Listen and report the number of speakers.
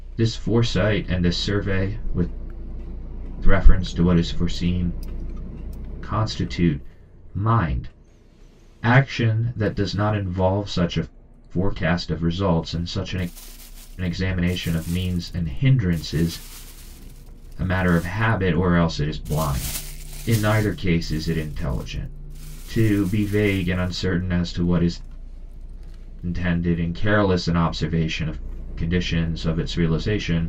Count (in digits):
1